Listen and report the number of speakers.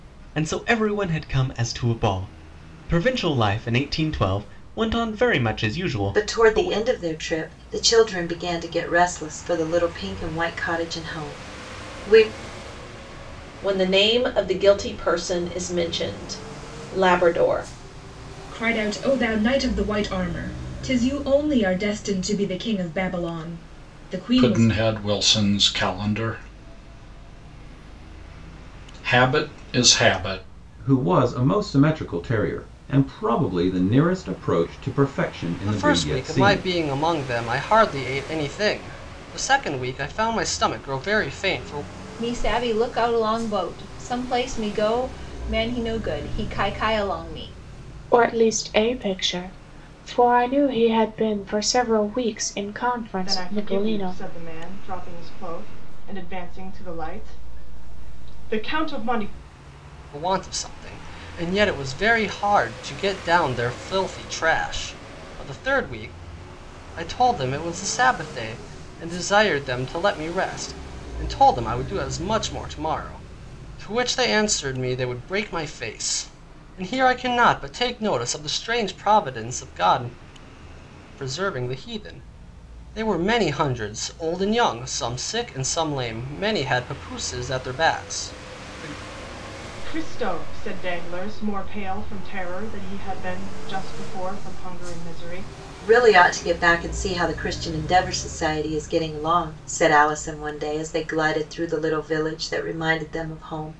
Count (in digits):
10